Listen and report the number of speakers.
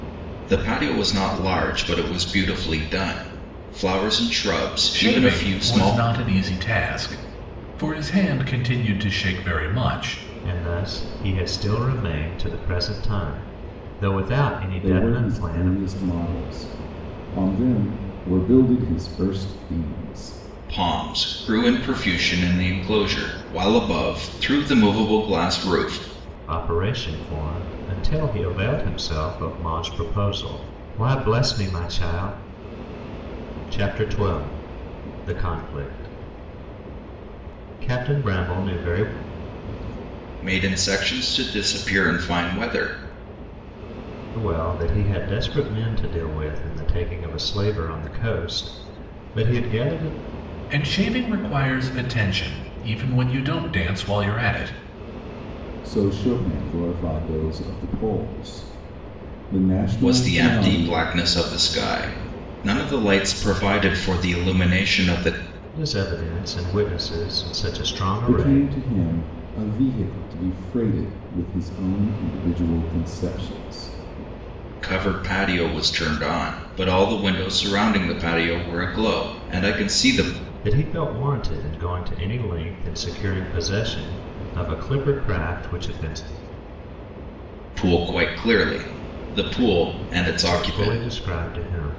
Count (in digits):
4